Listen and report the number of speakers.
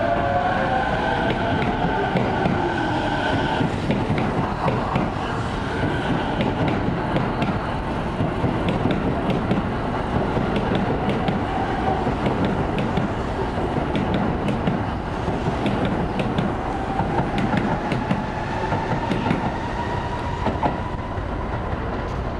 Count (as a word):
zero